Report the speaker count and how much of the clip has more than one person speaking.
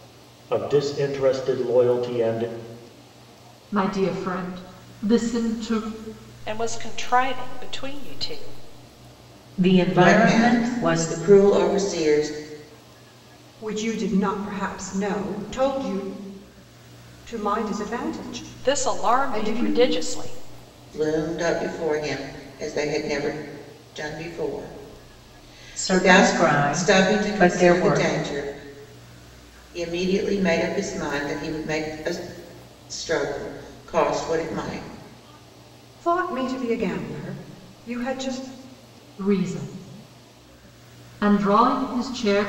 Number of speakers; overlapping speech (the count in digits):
6, about 10%